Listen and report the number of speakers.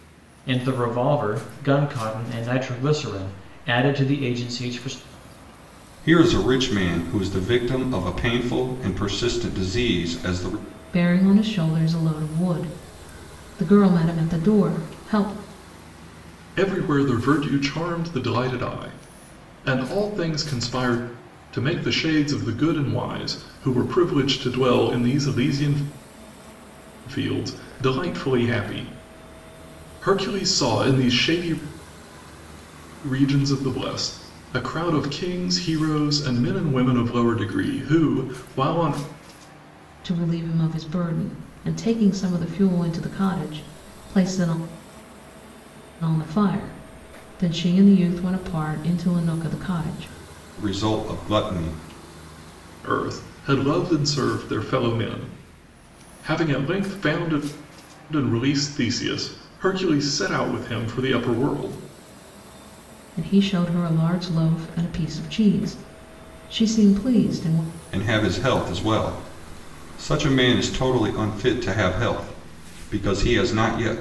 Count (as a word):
four